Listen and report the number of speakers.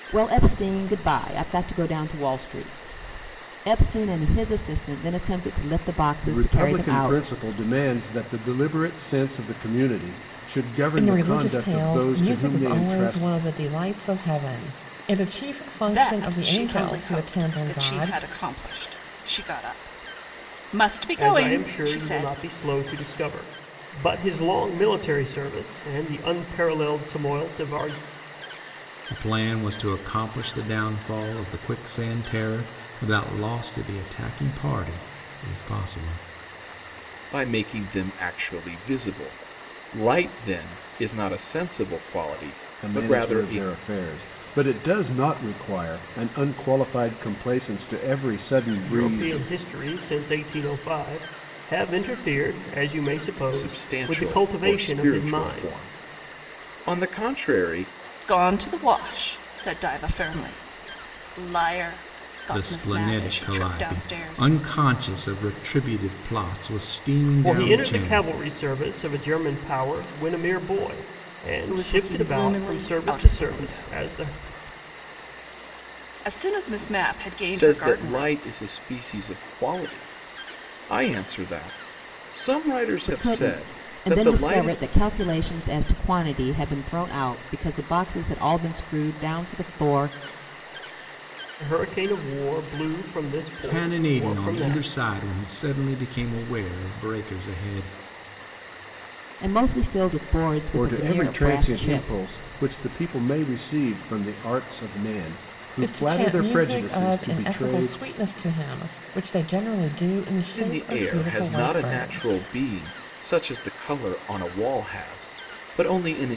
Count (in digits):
7